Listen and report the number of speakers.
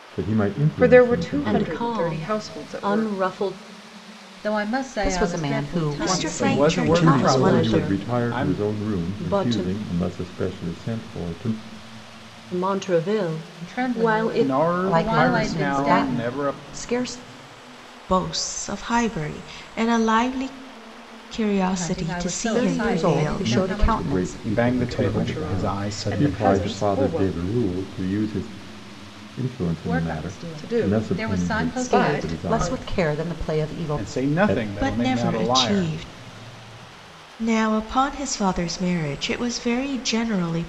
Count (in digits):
7